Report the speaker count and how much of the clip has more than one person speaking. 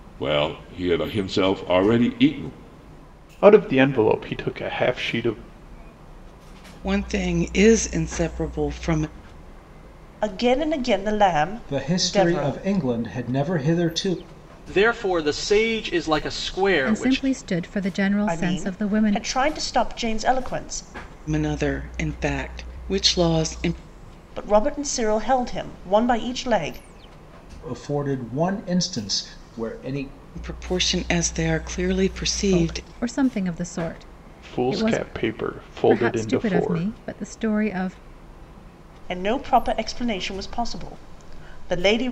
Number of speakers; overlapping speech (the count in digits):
7, about 11%